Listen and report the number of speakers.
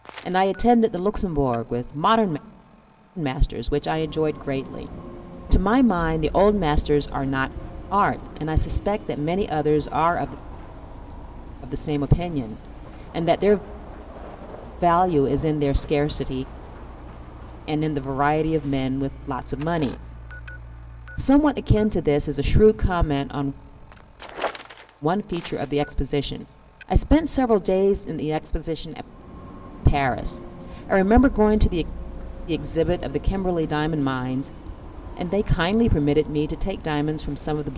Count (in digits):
1